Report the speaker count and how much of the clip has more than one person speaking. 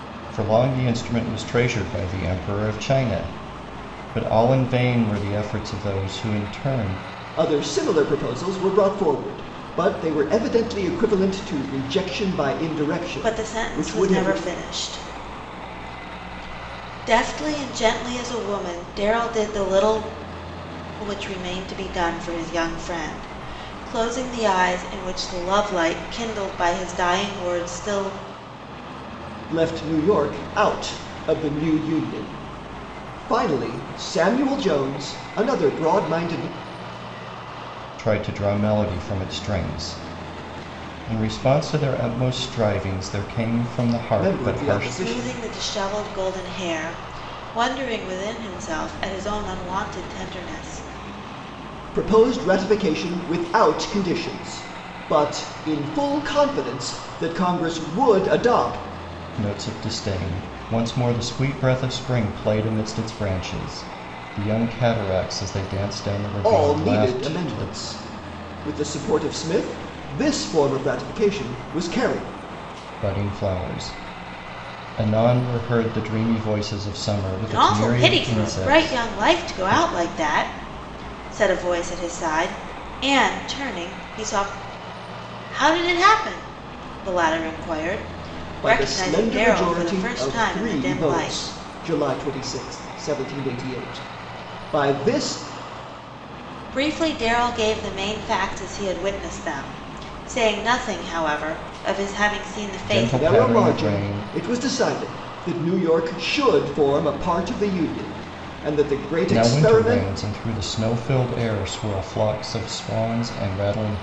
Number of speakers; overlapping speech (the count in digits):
3, about 10%